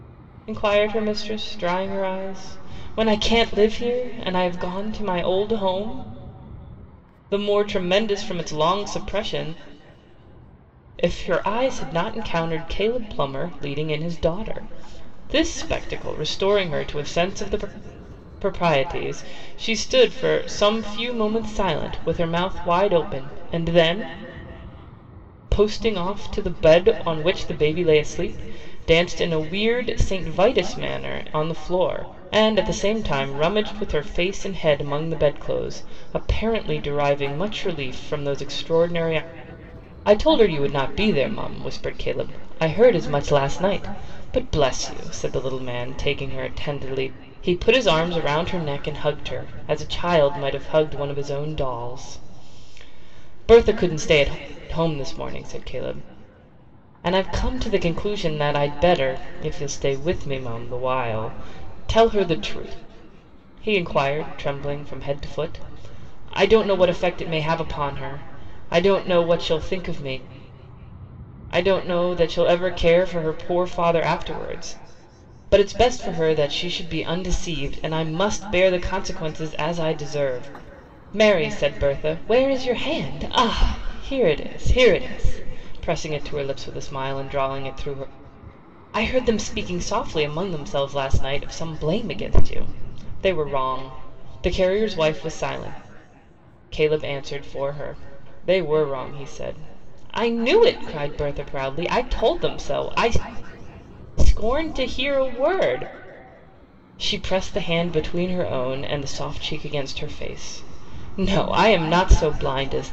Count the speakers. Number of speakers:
1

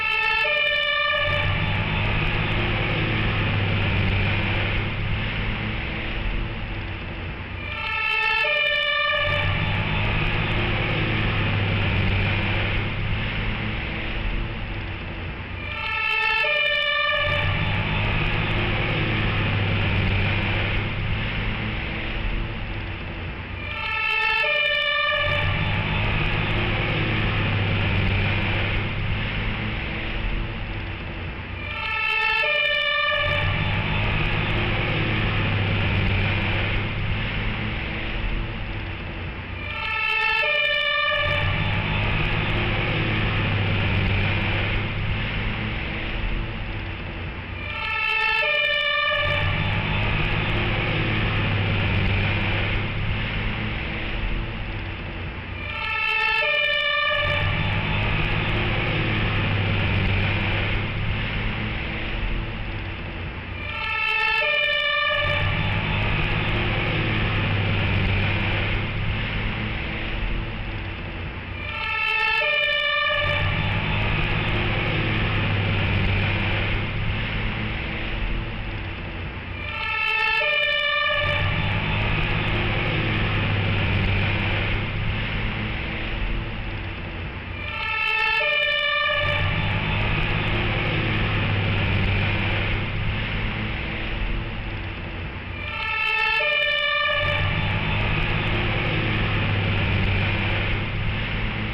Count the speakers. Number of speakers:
0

